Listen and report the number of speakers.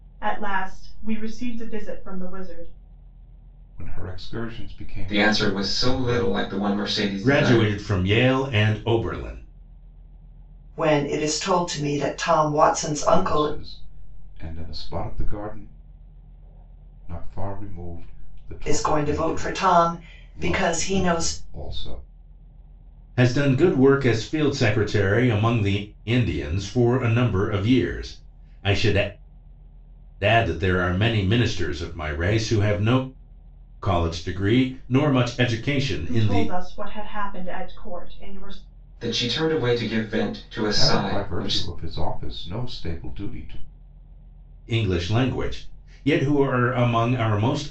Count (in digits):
5